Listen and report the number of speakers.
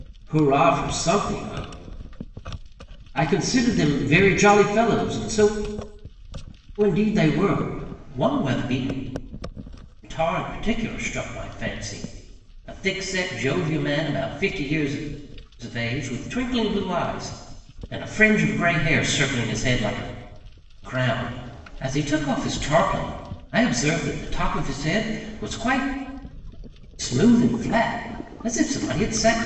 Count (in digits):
1